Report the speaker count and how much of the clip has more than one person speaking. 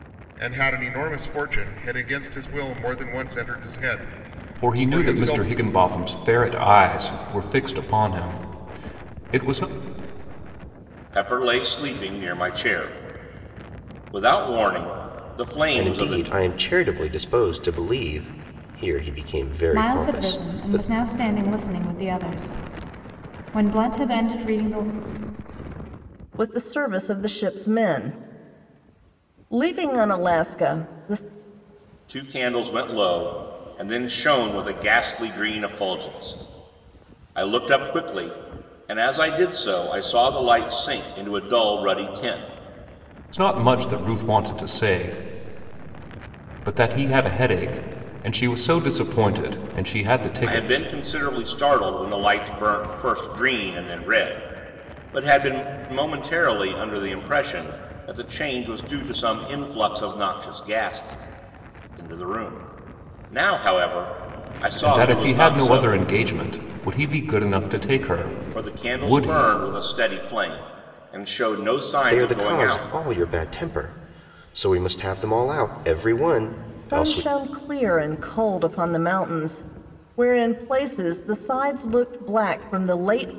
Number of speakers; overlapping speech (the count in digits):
6, about 8%